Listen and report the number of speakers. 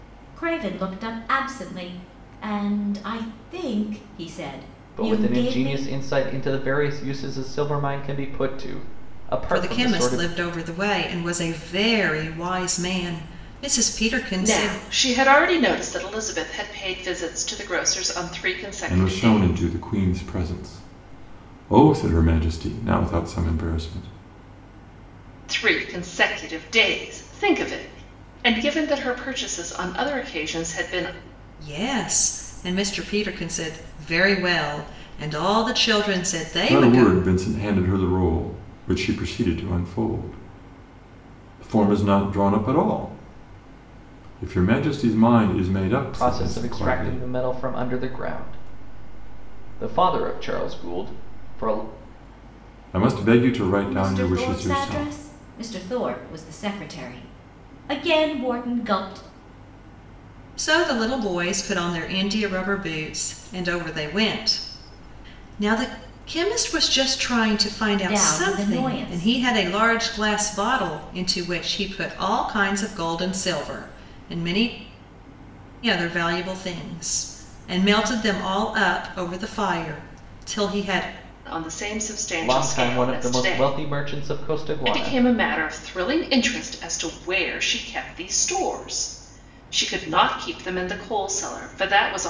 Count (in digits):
5